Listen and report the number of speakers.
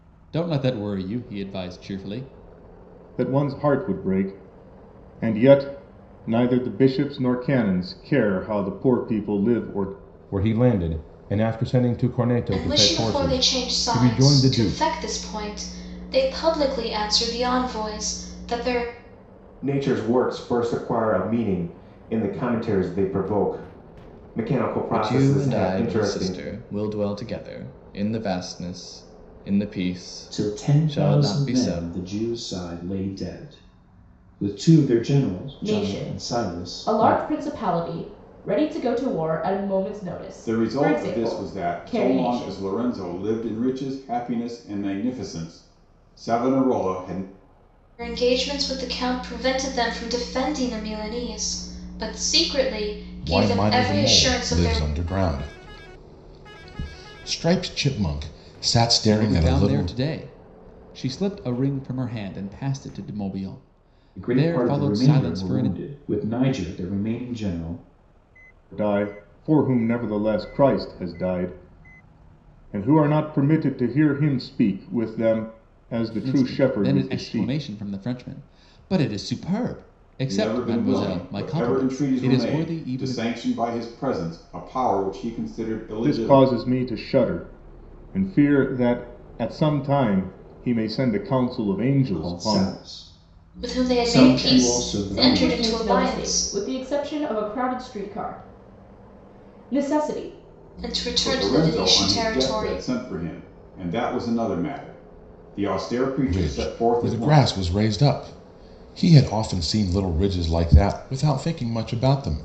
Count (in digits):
9